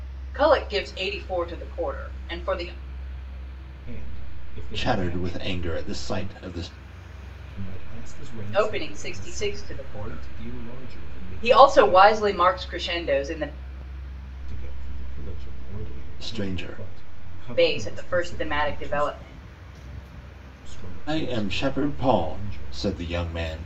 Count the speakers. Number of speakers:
3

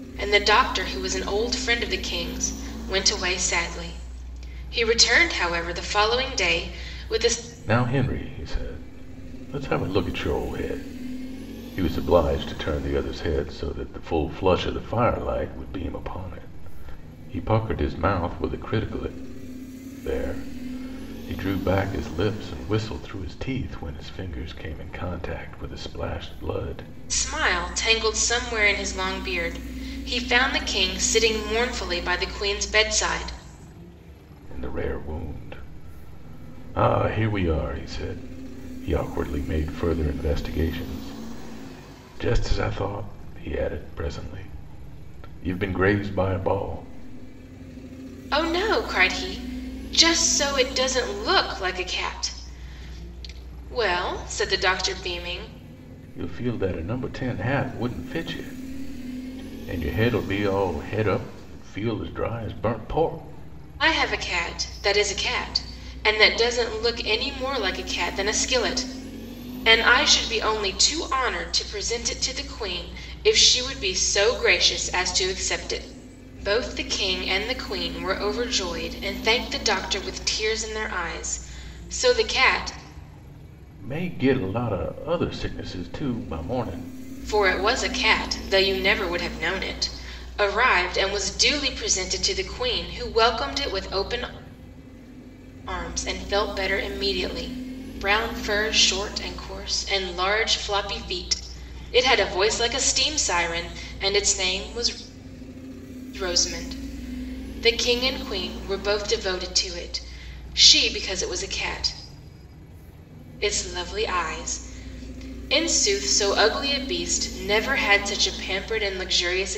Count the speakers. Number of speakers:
2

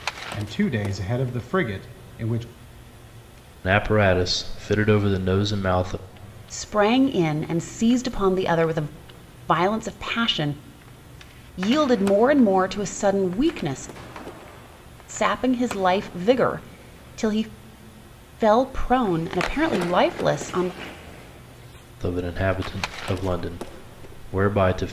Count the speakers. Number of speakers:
3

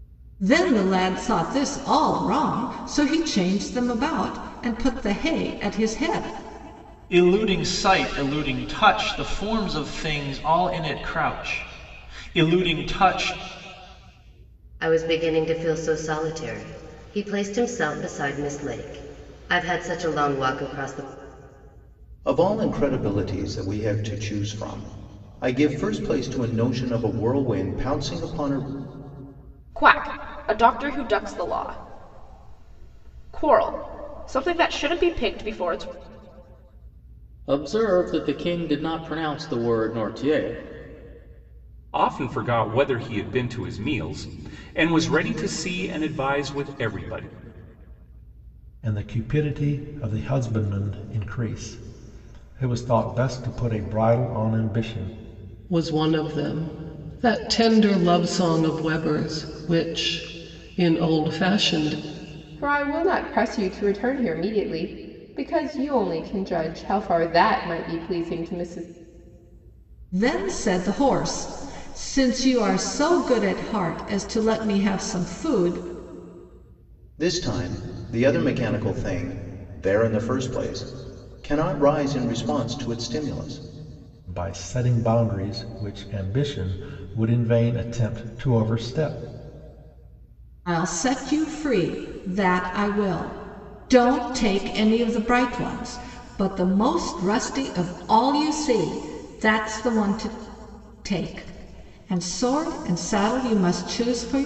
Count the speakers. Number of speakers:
10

